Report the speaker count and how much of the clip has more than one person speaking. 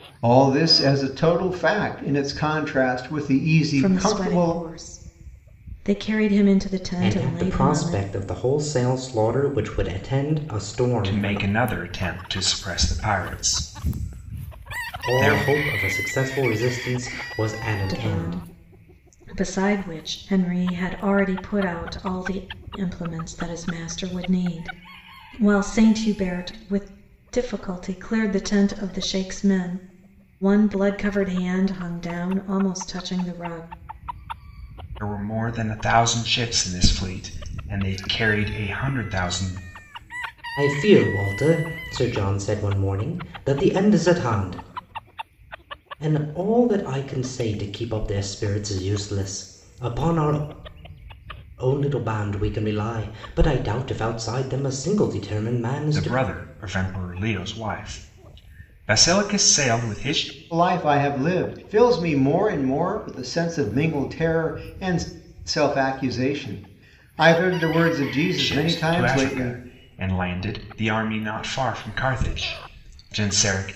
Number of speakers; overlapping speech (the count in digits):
4, about 7%